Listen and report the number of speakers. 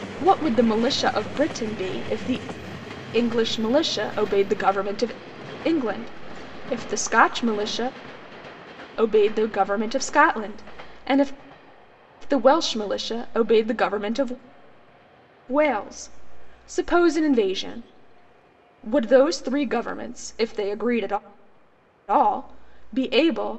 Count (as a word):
one